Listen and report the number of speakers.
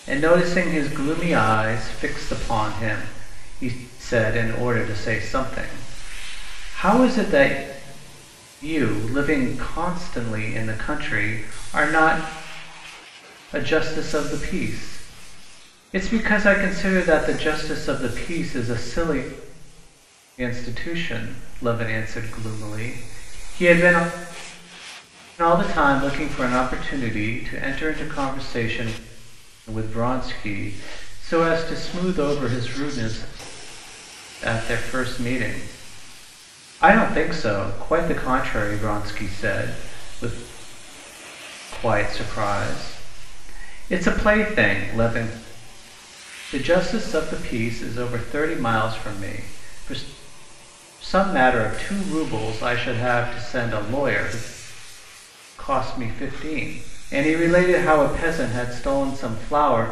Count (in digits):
1